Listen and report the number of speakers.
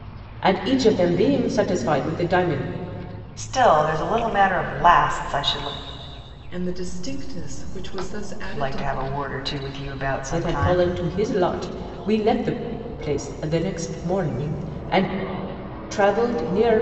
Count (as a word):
three